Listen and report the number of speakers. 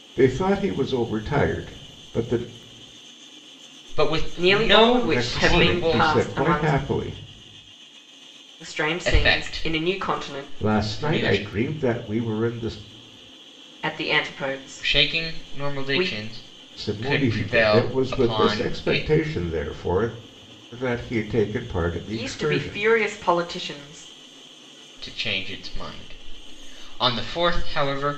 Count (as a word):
three